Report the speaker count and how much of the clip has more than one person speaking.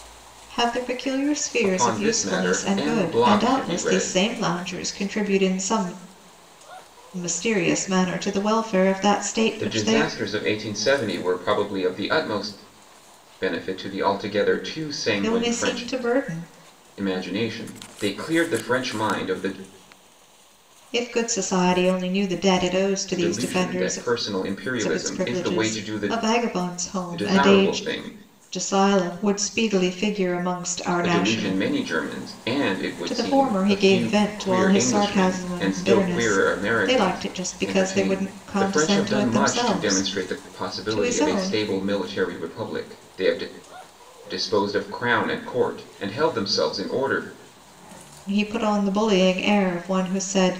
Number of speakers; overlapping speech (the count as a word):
two, about 31%